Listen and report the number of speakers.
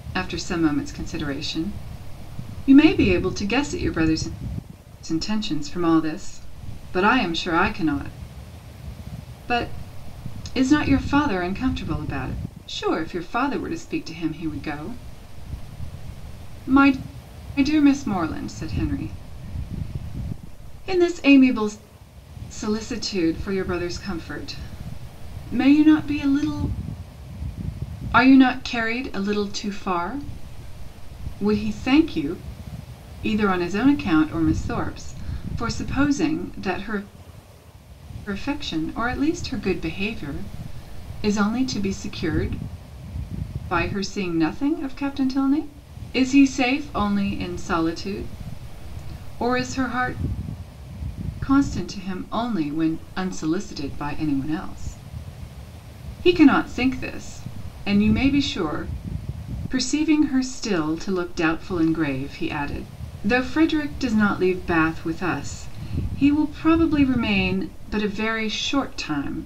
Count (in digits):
1